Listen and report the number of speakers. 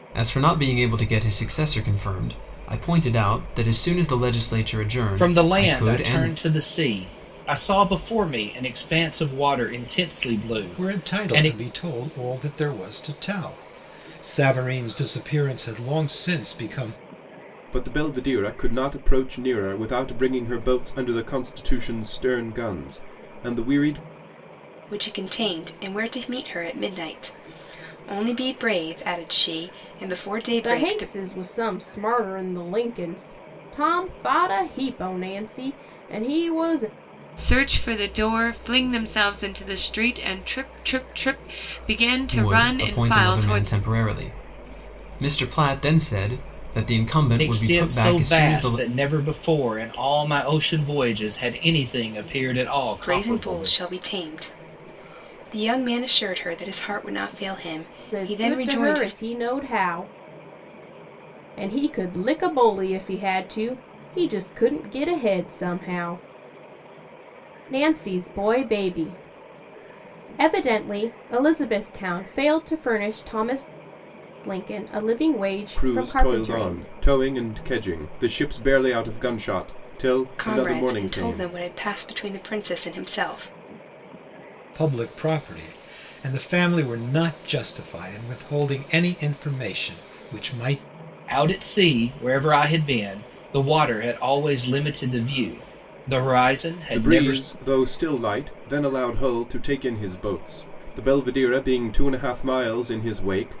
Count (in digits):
7